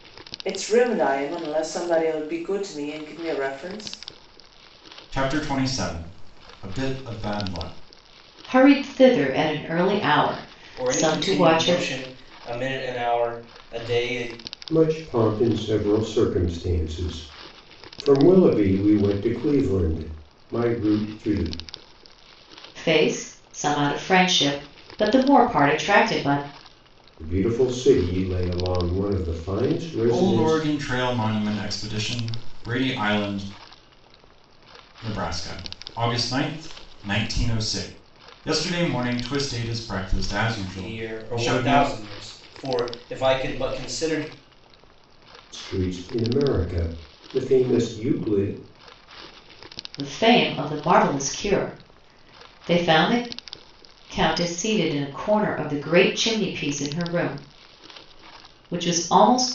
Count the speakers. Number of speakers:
5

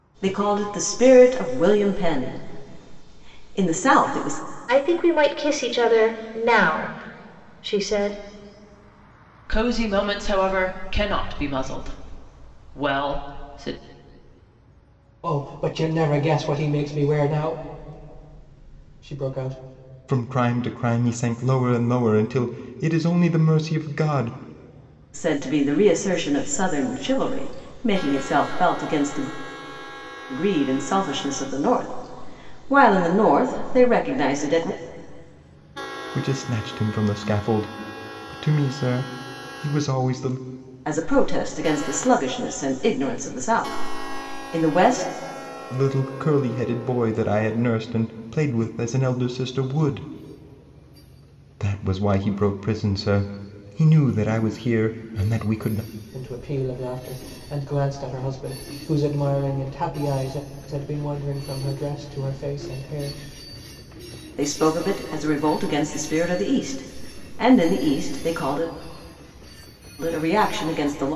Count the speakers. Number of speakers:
5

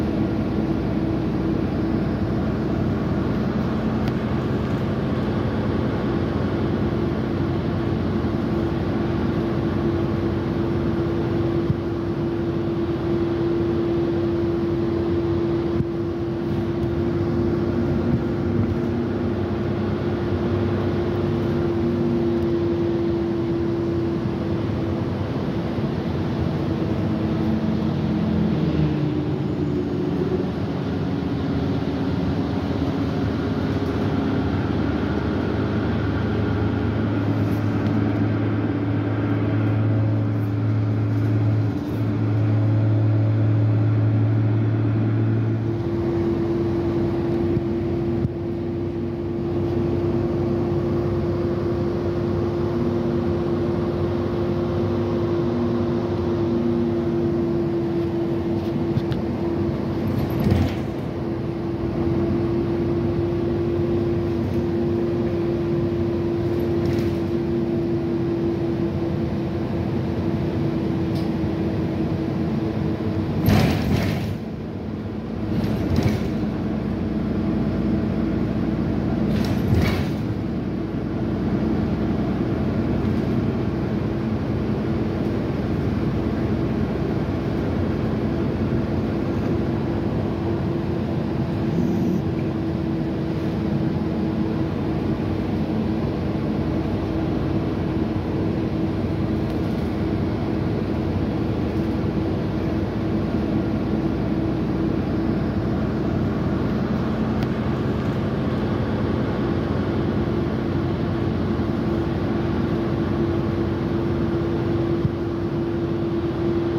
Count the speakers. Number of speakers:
0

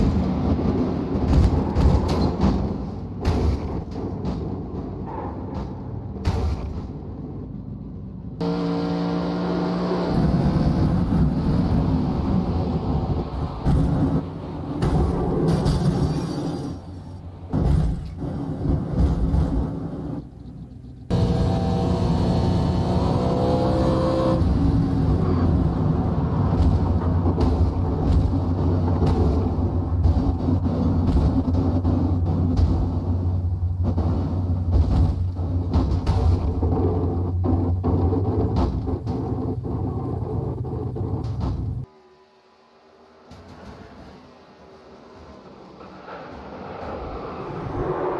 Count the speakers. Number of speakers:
0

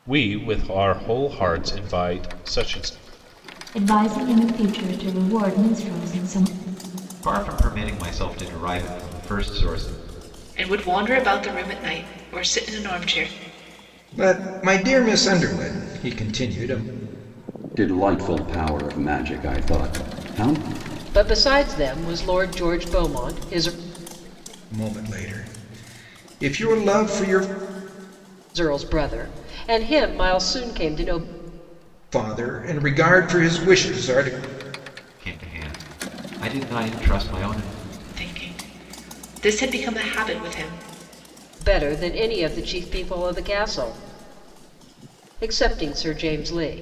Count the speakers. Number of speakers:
7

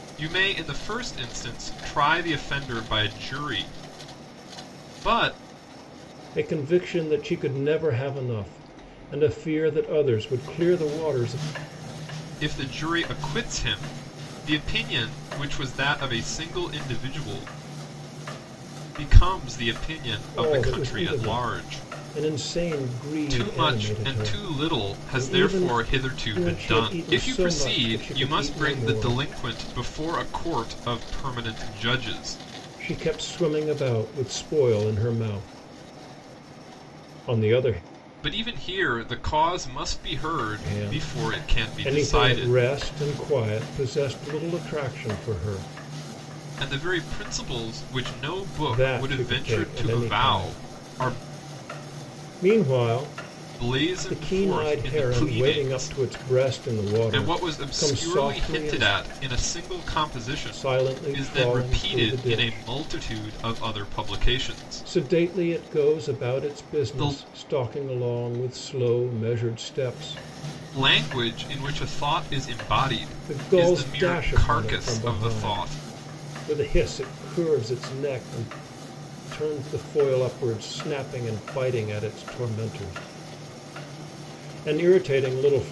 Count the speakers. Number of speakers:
2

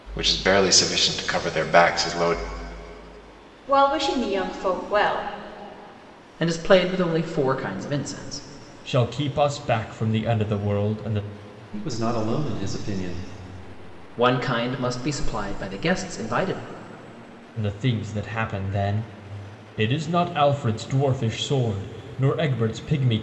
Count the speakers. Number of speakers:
5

